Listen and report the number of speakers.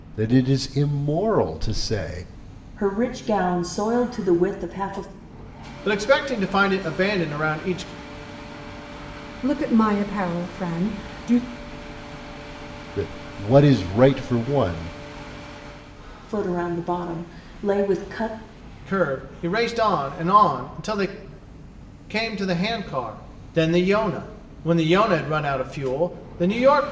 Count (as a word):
four